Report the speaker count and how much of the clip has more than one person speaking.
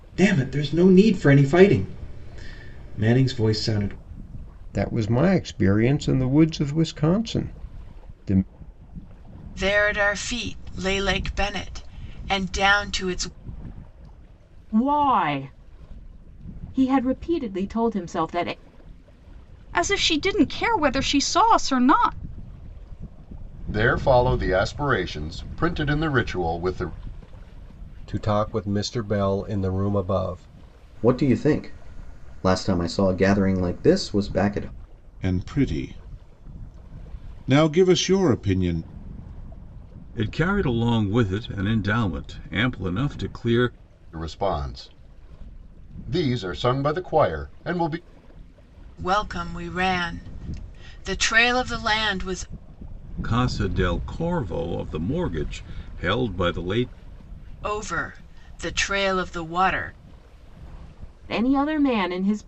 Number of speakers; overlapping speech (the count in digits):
10, no overlap